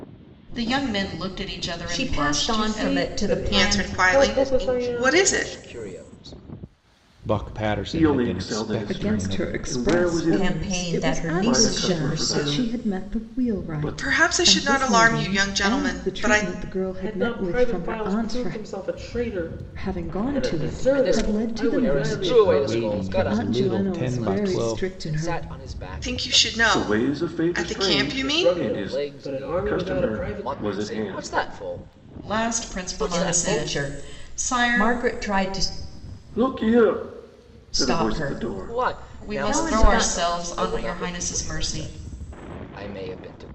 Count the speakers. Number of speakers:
eight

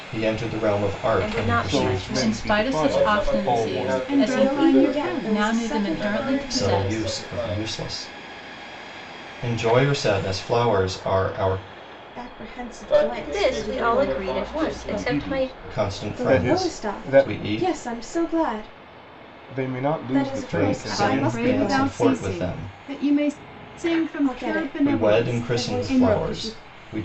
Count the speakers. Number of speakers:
seven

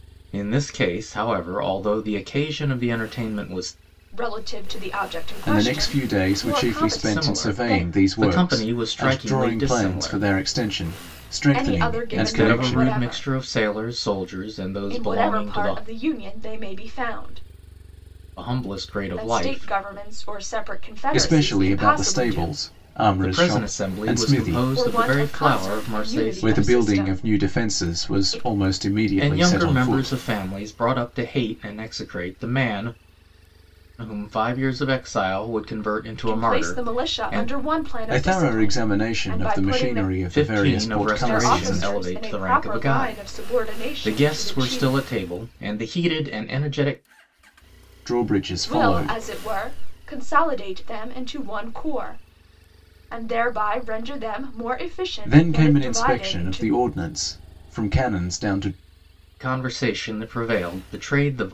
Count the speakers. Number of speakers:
three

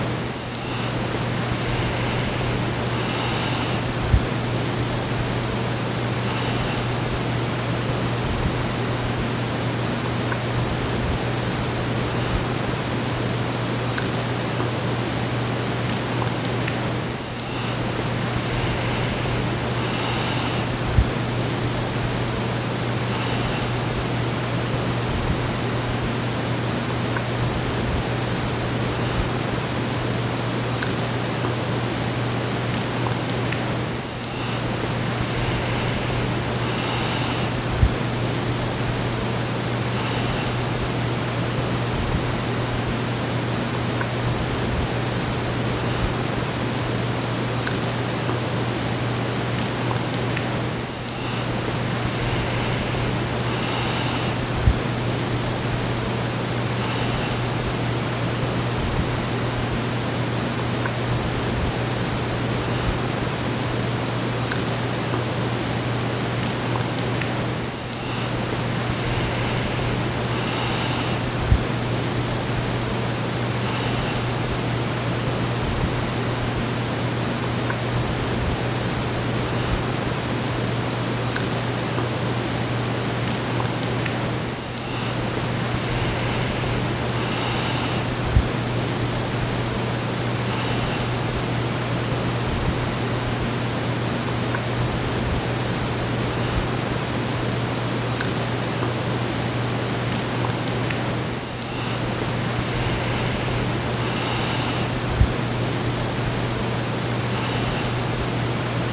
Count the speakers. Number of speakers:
zero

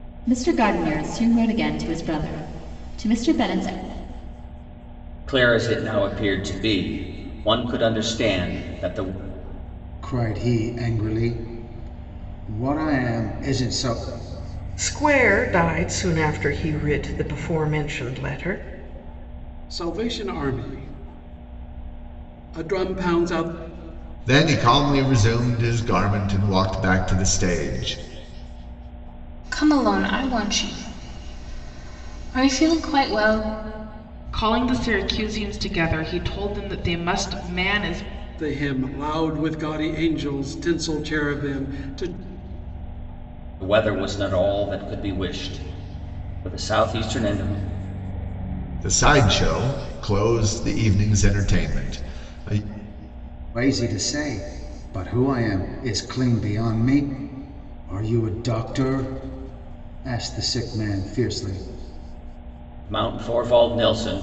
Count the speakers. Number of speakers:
eight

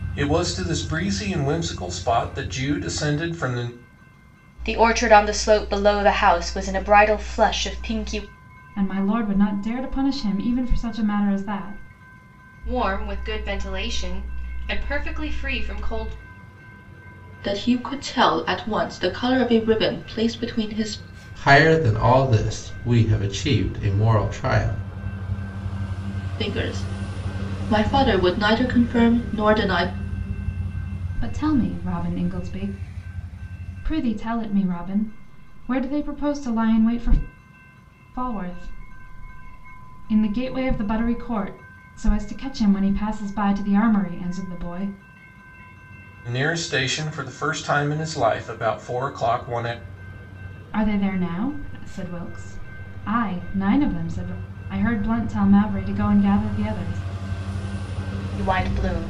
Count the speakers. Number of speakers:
six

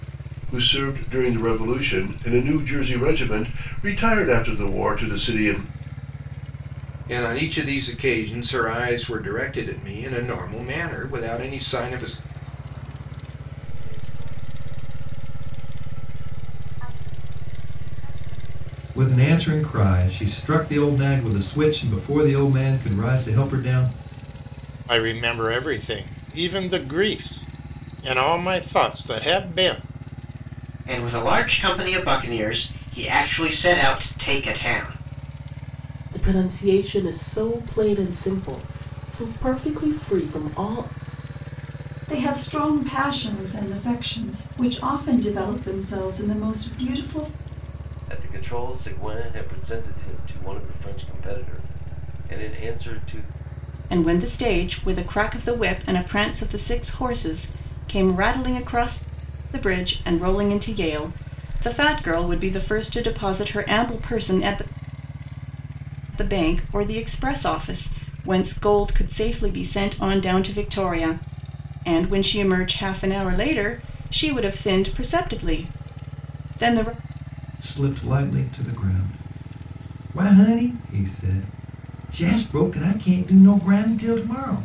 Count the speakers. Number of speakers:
ten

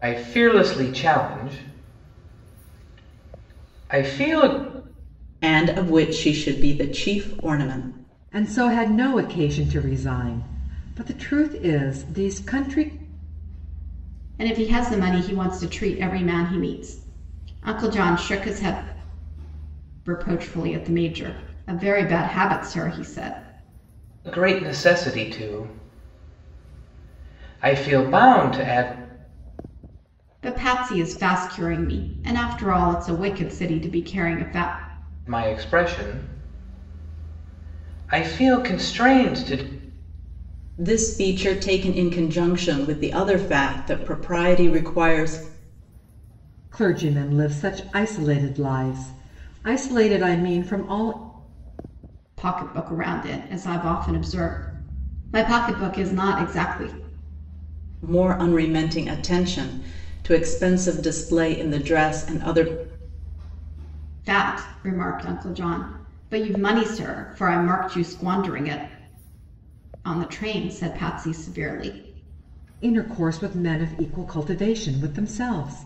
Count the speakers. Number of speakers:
four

